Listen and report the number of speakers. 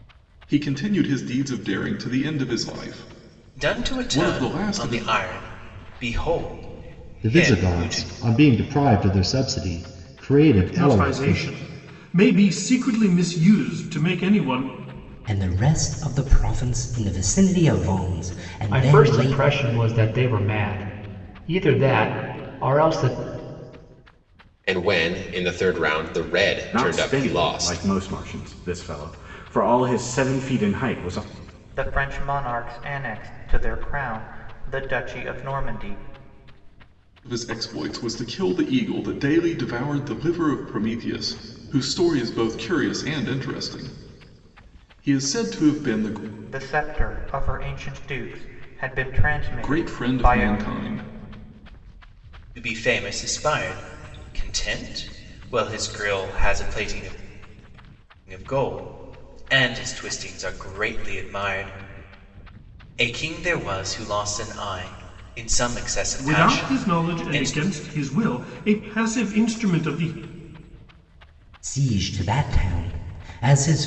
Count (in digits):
9